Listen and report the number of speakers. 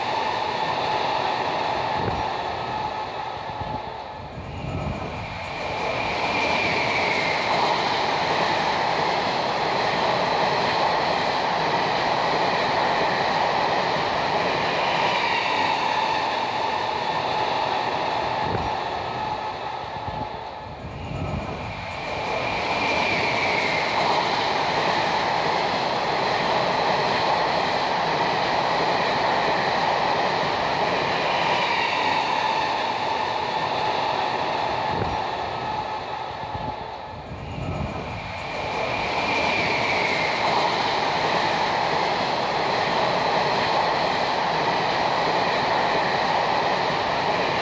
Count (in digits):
0